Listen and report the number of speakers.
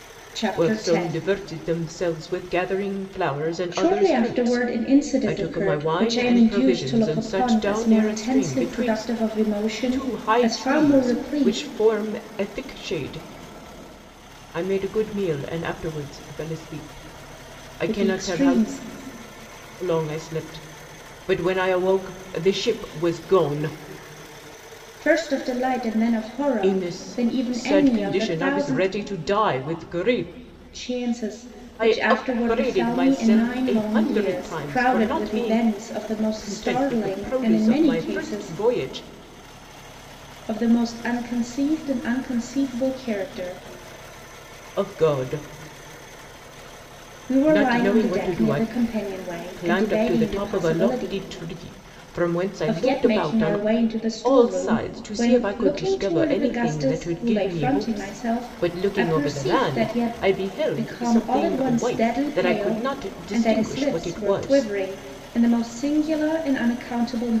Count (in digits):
2